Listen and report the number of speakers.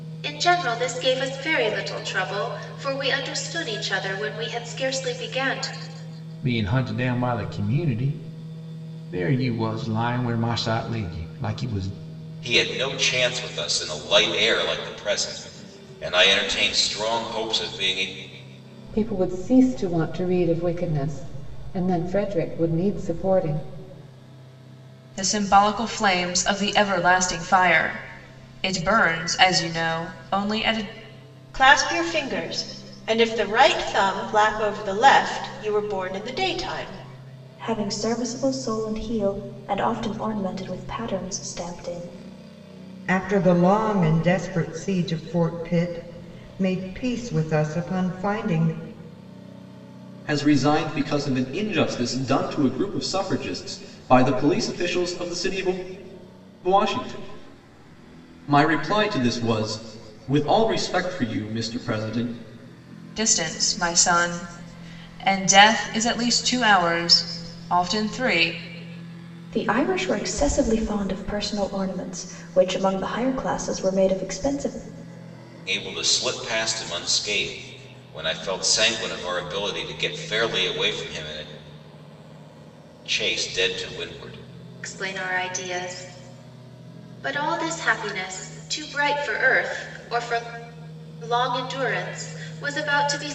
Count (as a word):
nine